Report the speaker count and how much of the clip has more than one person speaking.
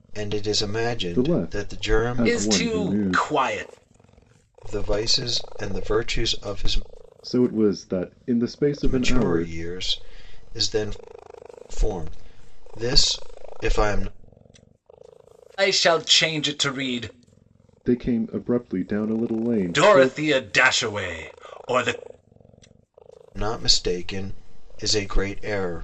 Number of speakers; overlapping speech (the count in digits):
3, about 13%